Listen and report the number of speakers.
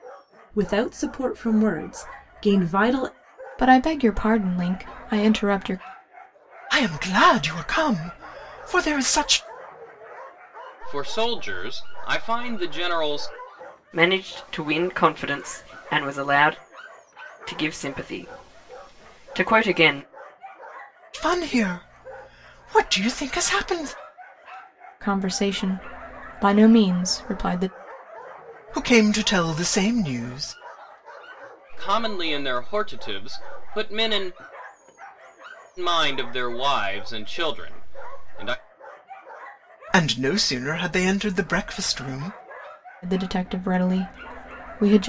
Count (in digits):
5